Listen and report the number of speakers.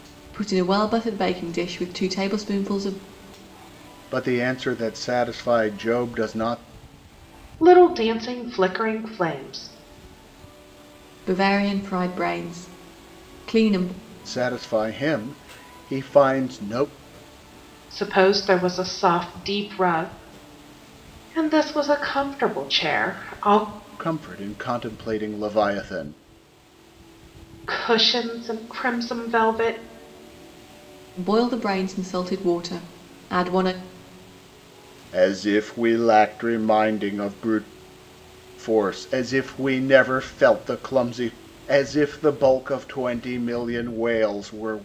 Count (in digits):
3